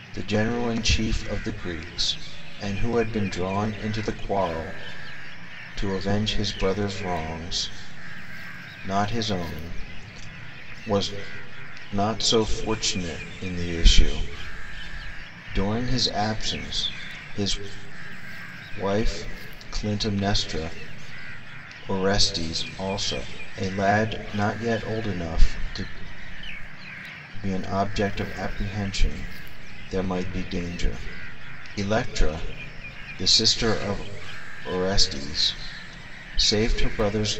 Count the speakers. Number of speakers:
1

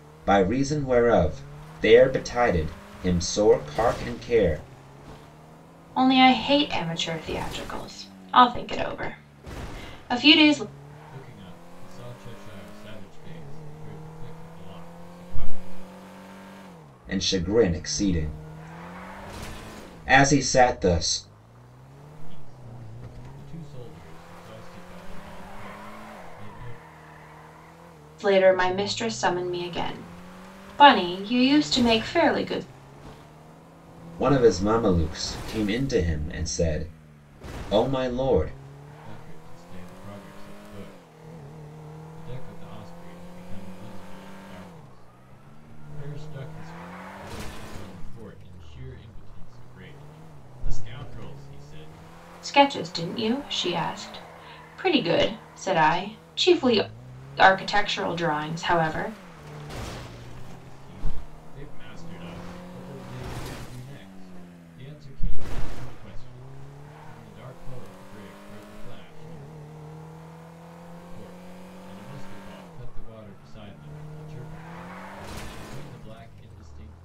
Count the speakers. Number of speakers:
3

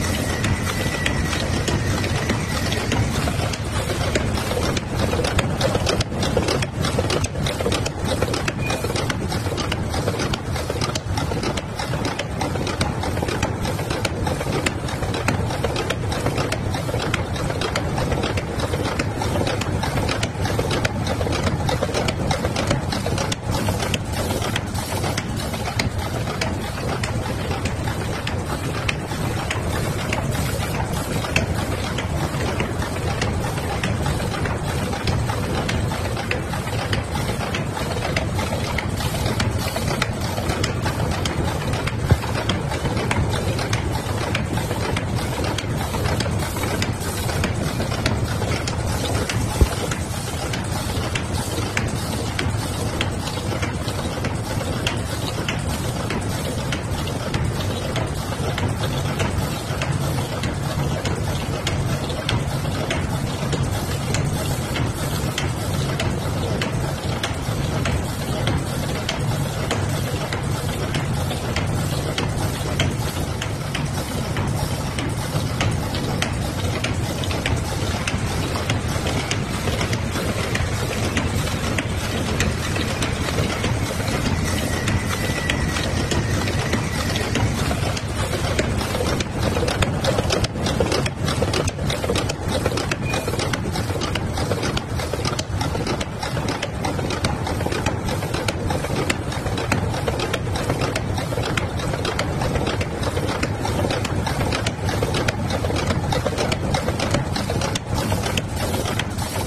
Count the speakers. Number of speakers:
0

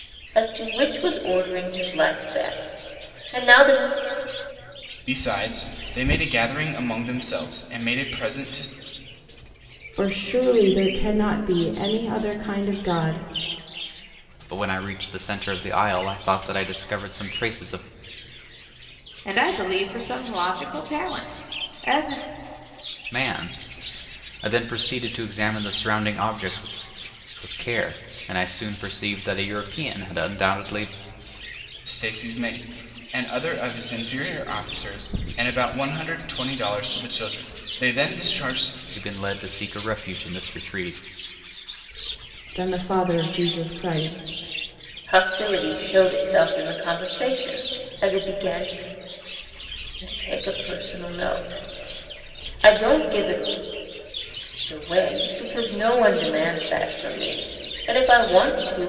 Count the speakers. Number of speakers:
5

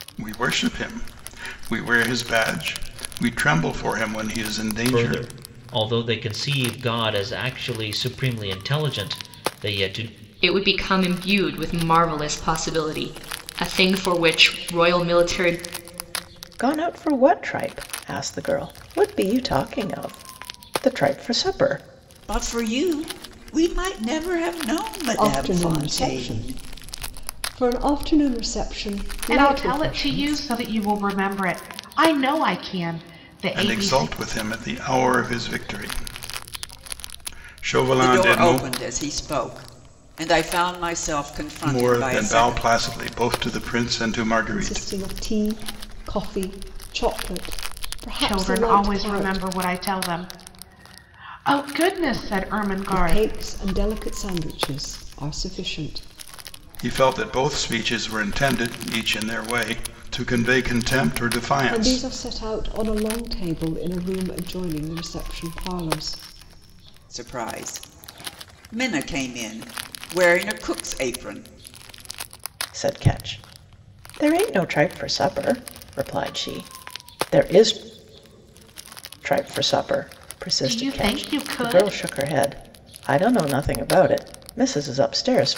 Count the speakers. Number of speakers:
7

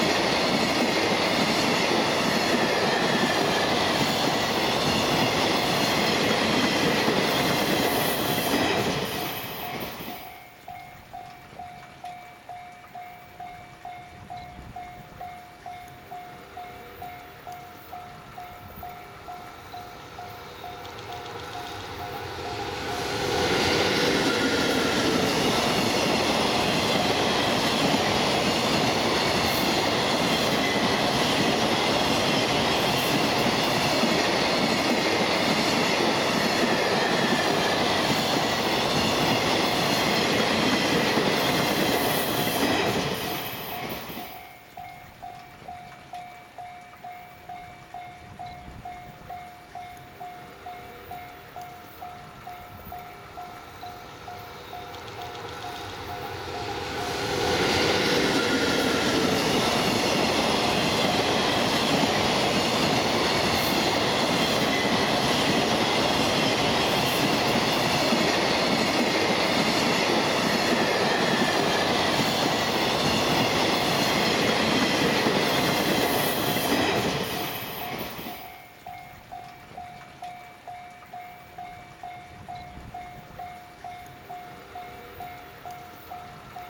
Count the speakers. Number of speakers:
0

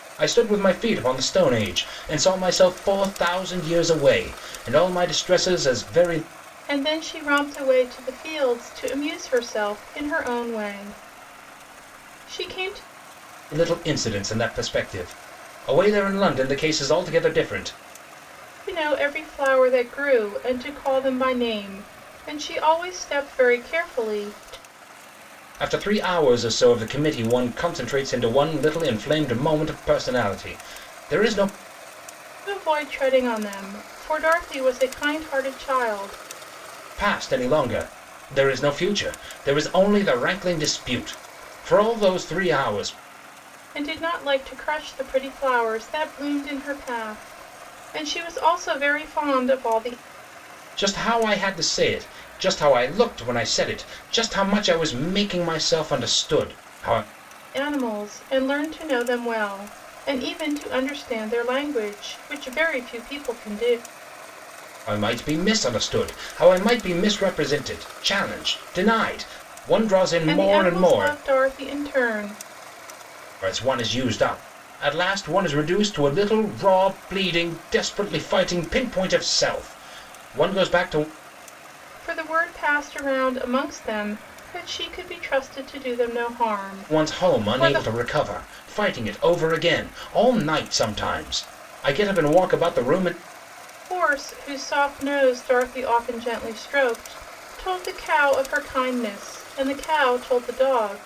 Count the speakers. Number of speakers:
2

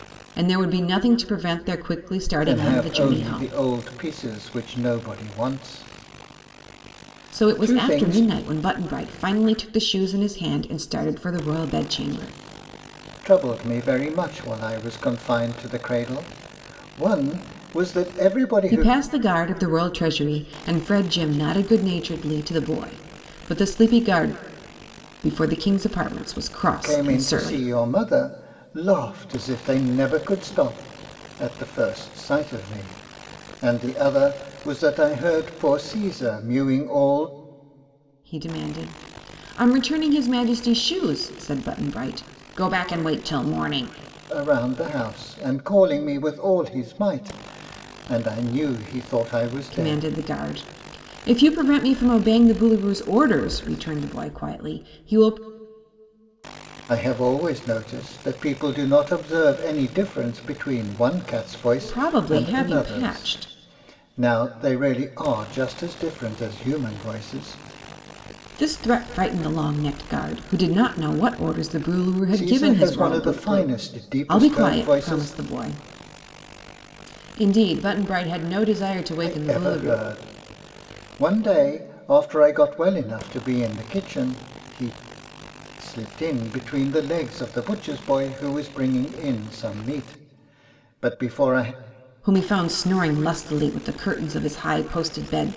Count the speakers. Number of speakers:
2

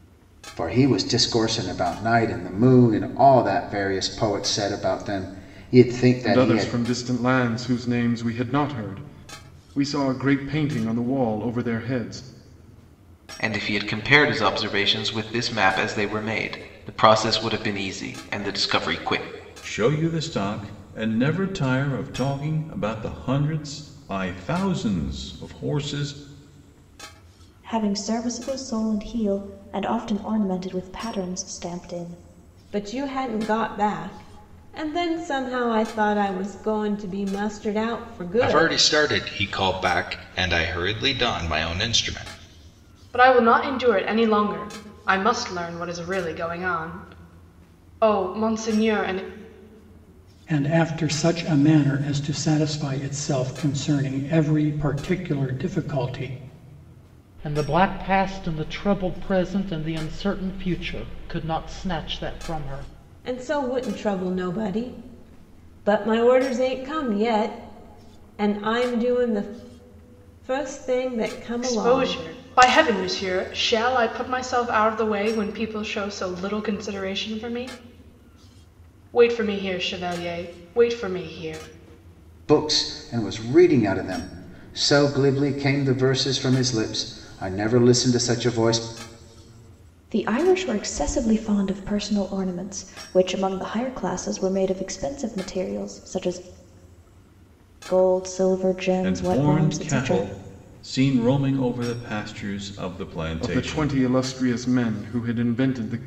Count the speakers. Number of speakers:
10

